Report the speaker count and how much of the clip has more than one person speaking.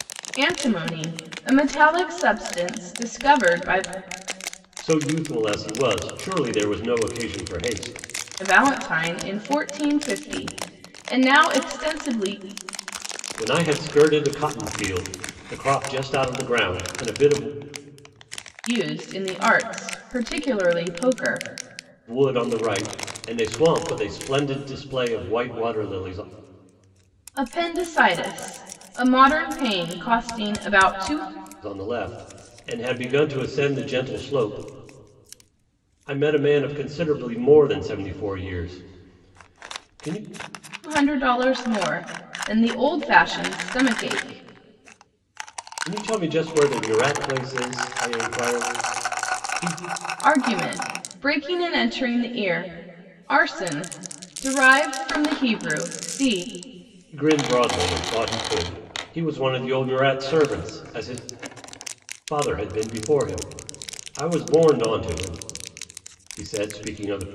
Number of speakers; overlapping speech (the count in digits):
2, no overlap